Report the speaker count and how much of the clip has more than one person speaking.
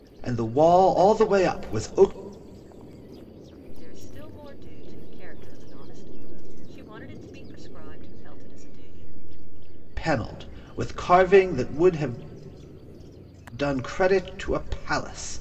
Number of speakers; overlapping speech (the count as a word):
two, no overlap